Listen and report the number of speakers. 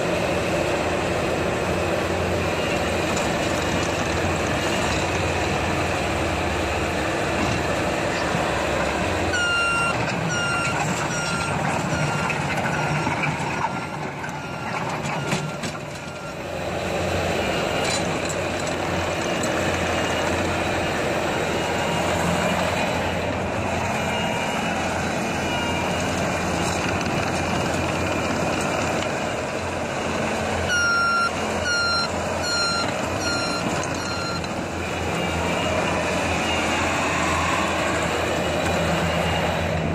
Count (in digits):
0